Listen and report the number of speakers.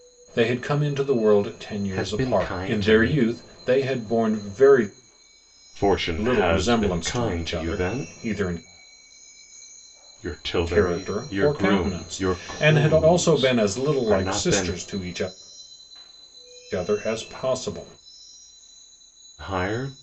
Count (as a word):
two